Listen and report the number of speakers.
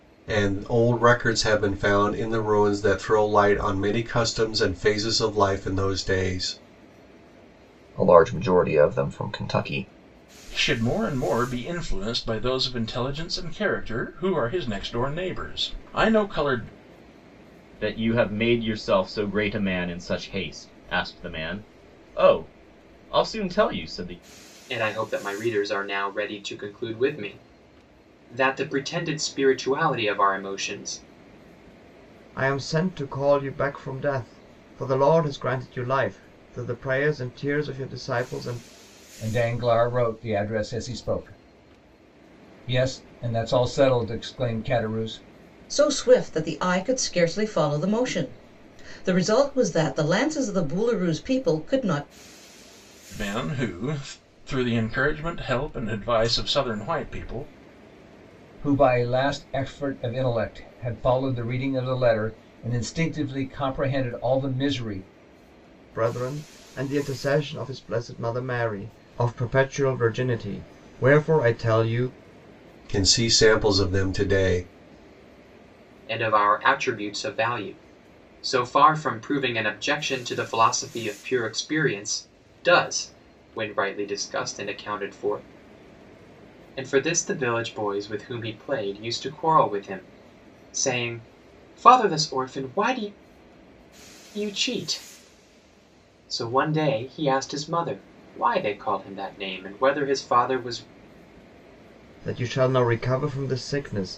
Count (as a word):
eight